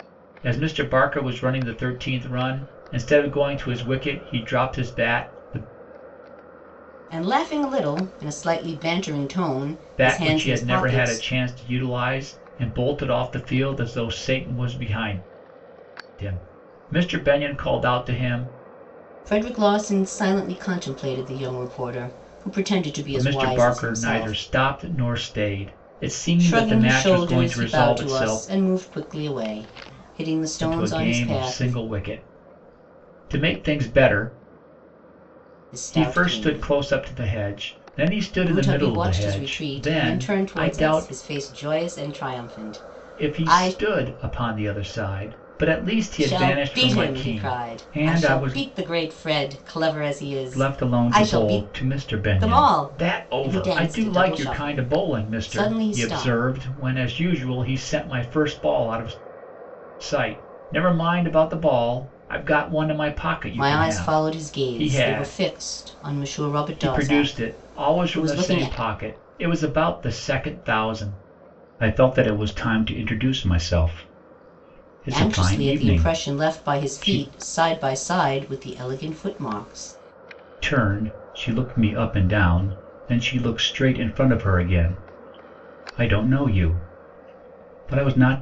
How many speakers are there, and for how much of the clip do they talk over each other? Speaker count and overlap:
two, about 27%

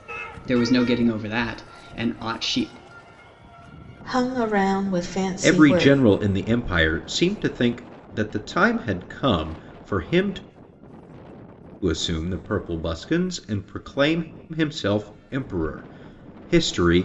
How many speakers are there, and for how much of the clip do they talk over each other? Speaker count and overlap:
three, about 4%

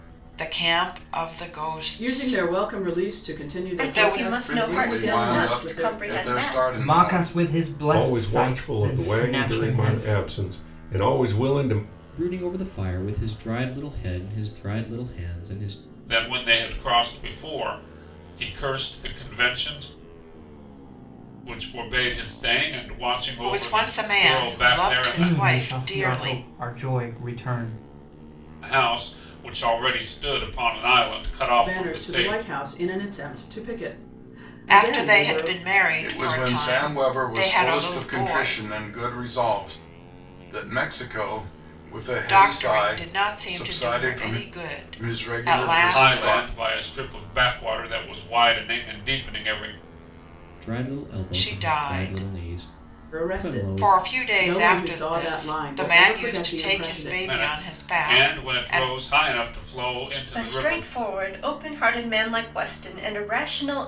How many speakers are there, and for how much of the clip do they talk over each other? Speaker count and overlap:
eight, about 42%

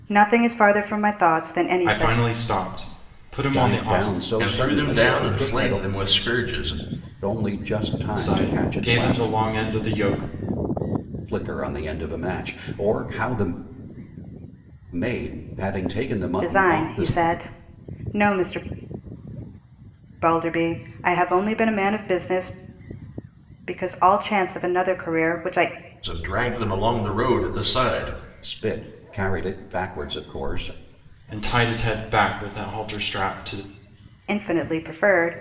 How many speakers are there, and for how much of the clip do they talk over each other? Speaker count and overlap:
four, about 13%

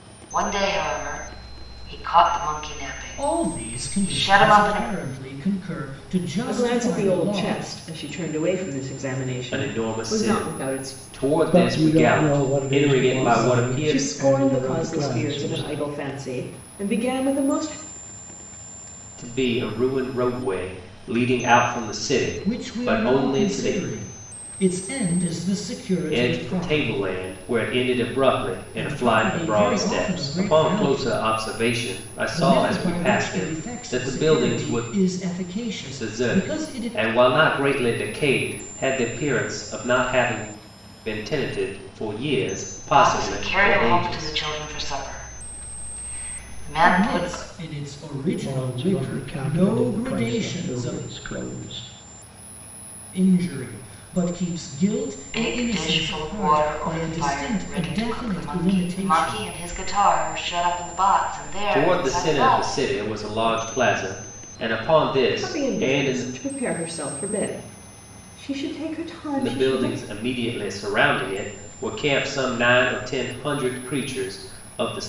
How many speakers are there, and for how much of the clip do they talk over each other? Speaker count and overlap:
five, about 39%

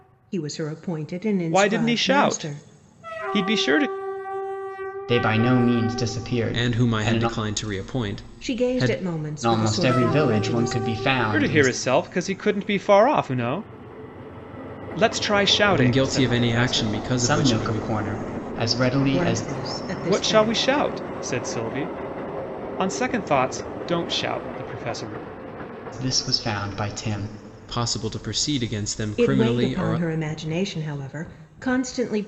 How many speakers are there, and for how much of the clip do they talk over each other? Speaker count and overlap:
four, about 26%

